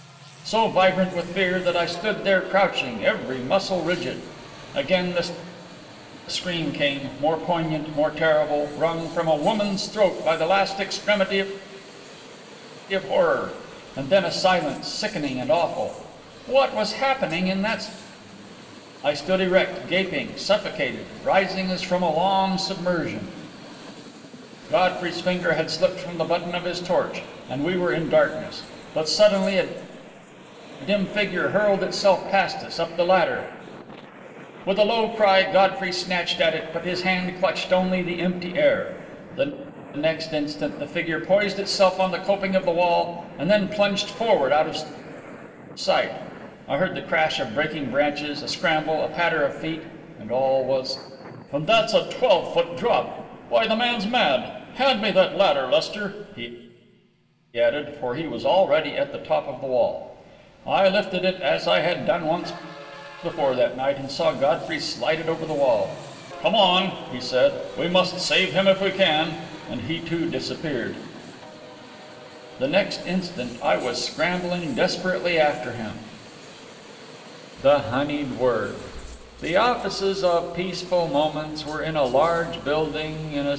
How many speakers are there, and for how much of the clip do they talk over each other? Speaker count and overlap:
1, no overlap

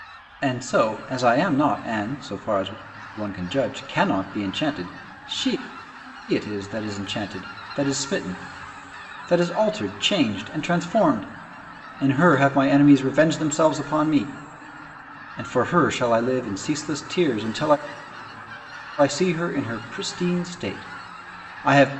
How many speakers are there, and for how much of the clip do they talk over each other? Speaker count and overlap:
1, no overlap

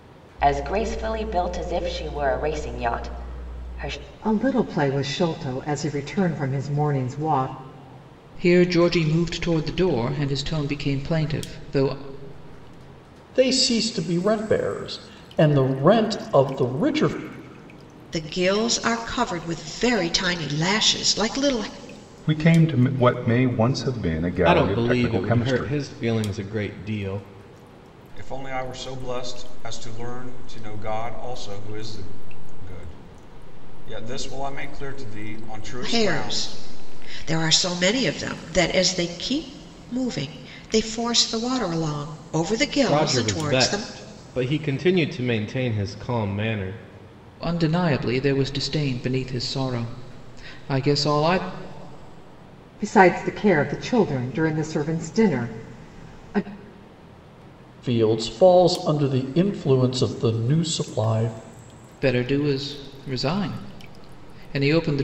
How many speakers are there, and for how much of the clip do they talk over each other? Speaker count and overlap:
8, about 5%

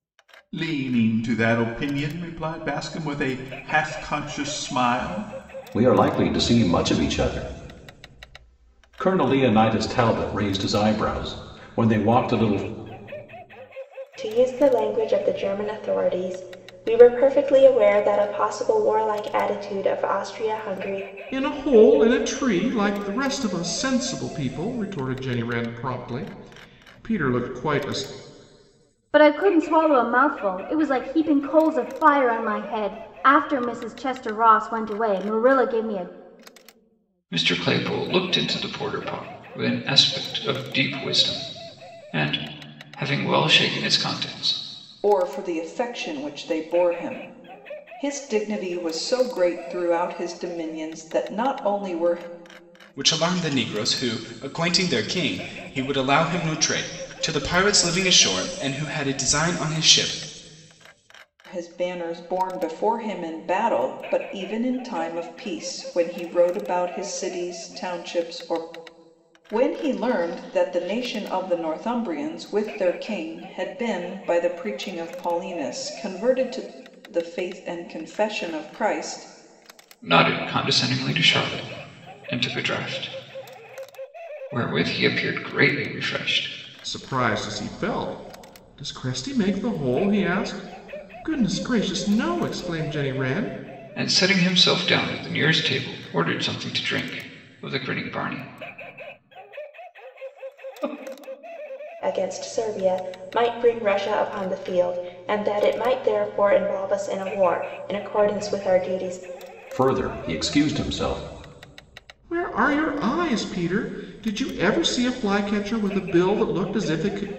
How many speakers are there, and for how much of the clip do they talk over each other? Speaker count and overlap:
8, no overlap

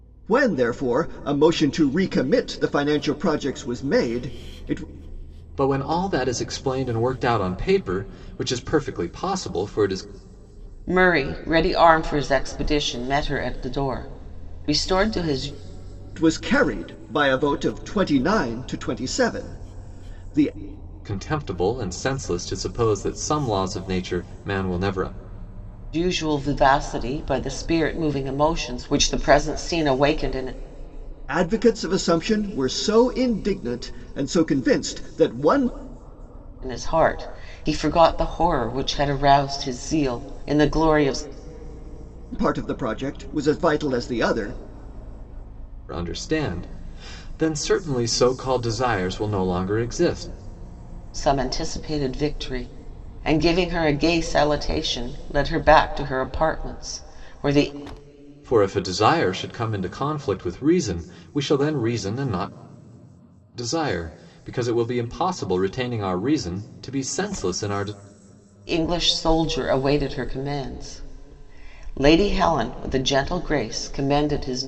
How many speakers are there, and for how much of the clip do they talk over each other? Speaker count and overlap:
3, no overlap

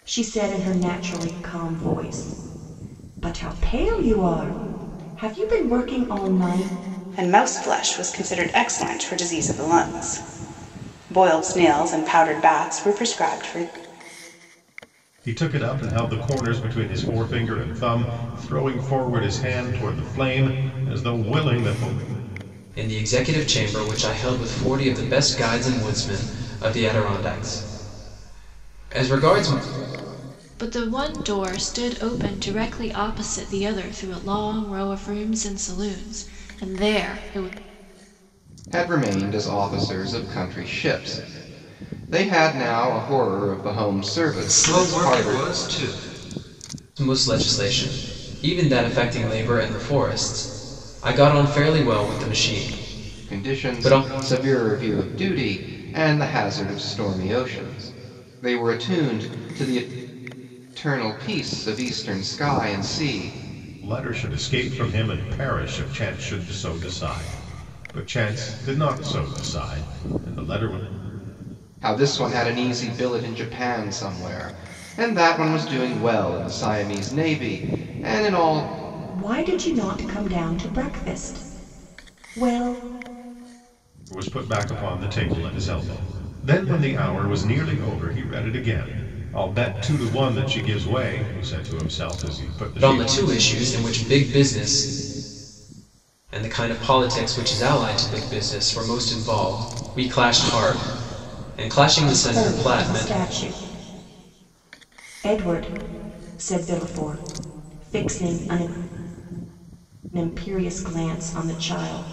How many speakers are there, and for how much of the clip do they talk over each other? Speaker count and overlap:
7, about 3%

